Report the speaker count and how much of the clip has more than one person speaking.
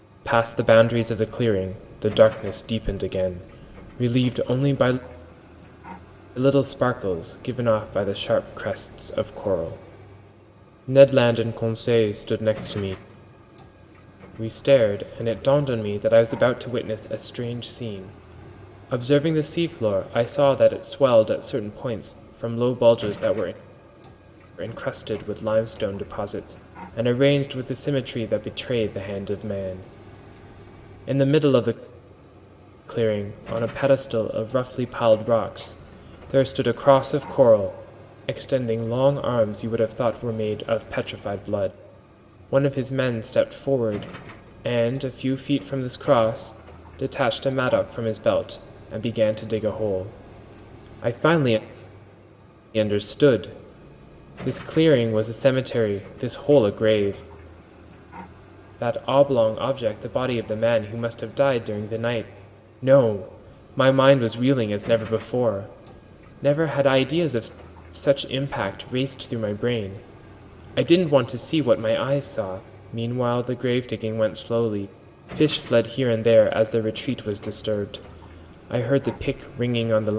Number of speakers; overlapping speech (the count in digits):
1, no overlap